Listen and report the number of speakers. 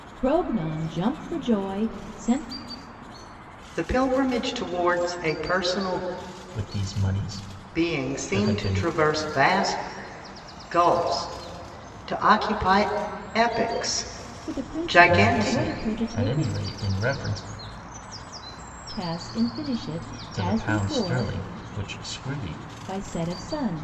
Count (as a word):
three